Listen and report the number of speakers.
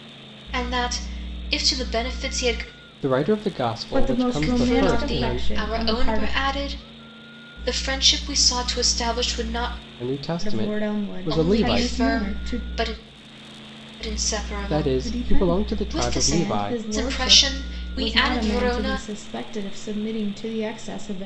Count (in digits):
3